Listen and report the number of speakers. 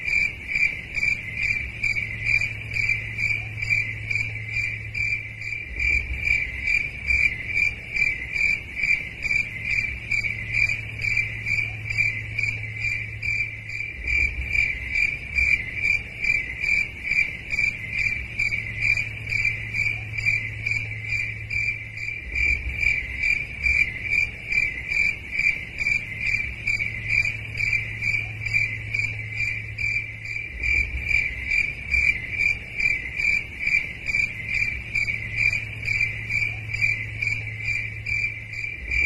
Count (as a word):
zero